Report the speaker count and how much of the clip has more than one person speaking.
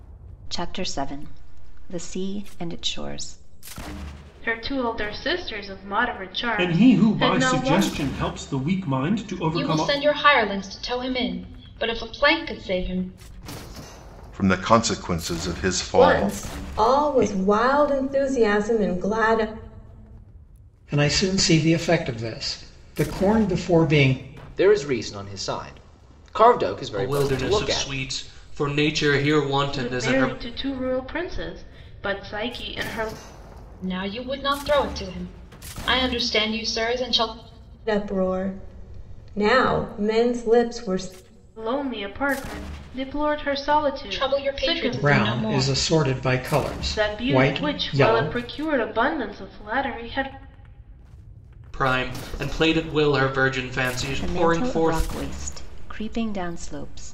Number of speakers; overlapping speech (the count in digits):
9, about 16%